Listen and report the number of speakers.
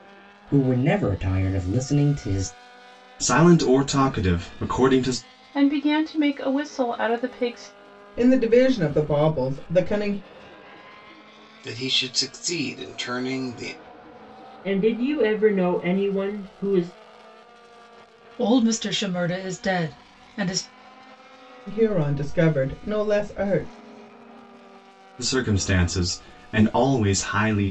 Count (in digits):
7